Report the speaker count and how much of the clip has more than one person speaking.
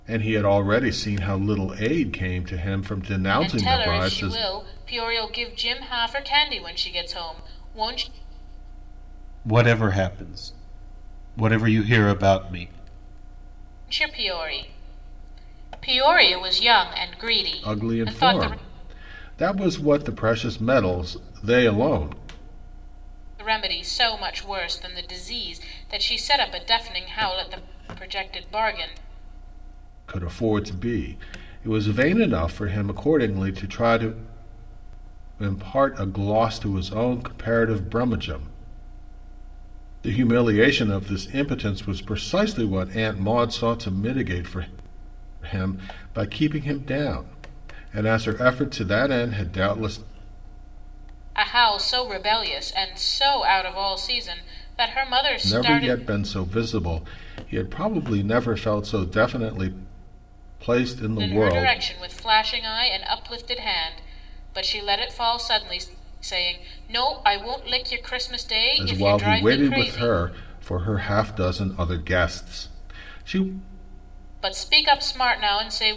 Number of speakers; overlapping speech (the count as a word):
three, about 6%